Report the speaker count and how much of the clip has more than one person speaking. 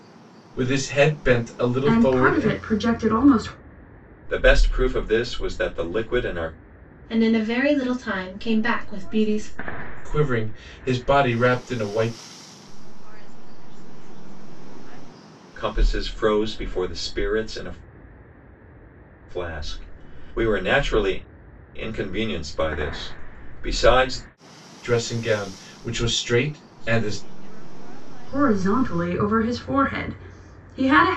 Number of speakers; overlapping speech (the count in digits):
5, about 12%